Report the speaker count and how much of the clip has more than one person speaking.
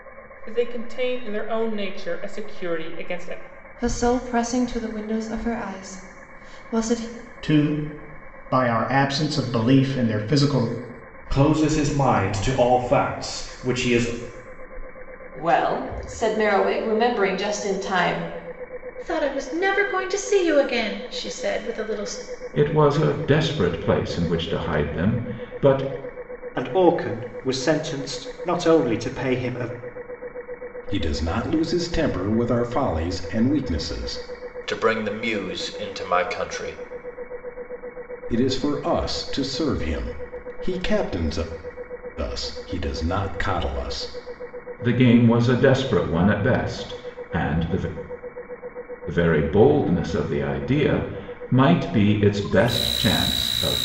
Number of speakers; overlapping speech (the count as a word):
ten, no overlap